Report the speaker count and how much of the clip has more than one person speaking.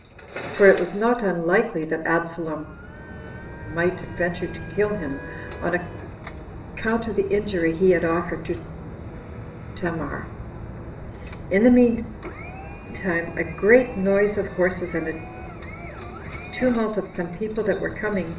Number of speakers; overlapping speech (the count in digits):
1, no overlap